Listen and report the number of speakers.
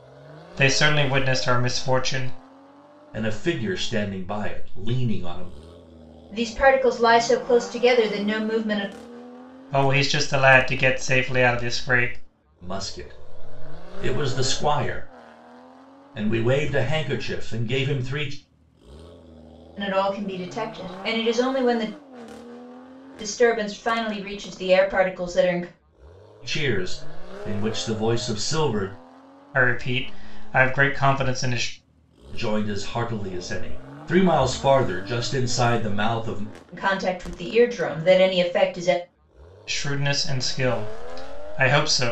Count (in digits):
3